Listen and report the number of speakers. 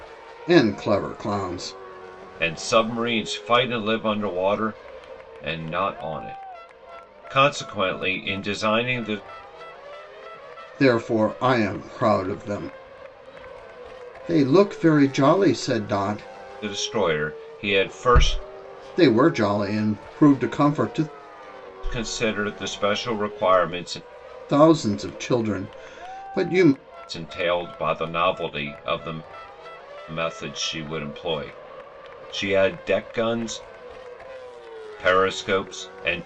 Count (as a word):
two